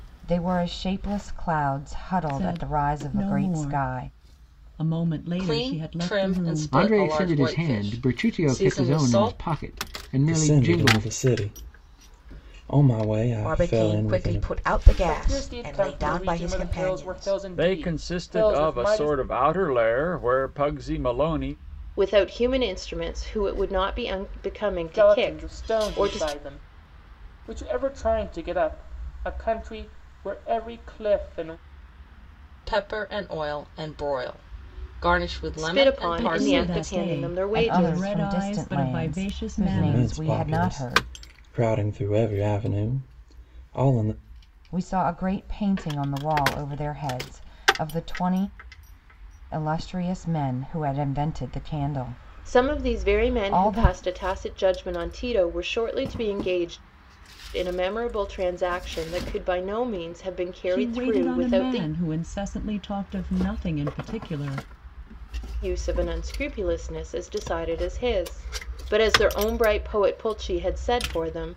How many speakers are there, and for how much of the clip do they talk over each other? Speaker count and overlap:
9, about 31%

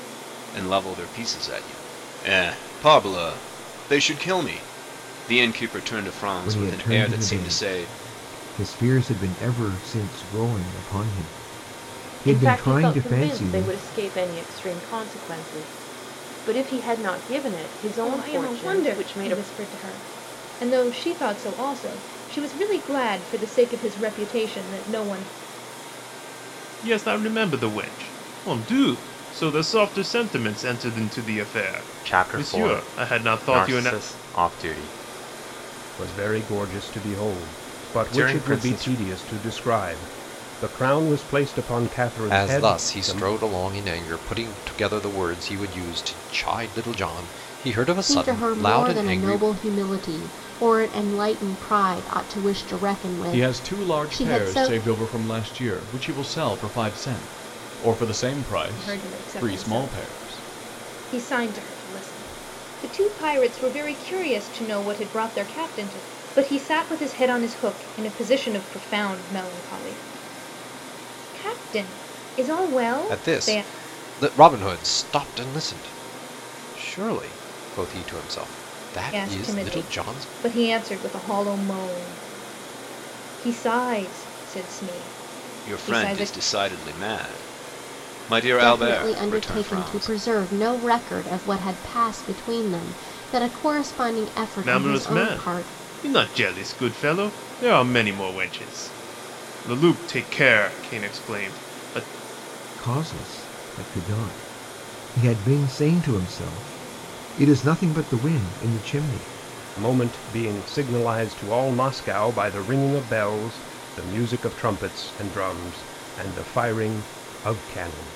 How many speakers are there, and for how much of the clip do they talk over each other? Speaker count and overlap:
10, about 17%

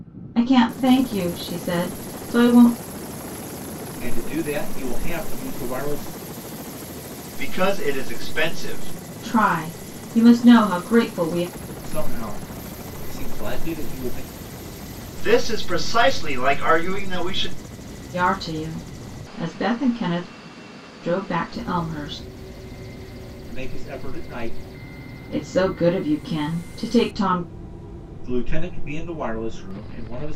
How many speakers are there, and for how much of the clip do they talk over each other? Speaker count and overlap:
3, no overlap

